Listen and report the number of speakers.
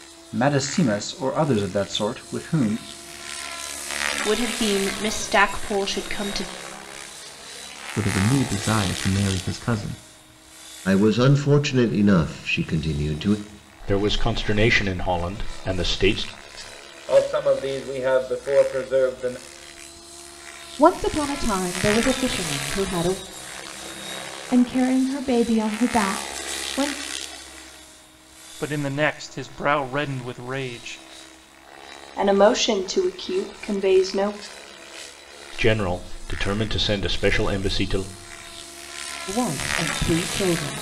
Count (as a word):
ten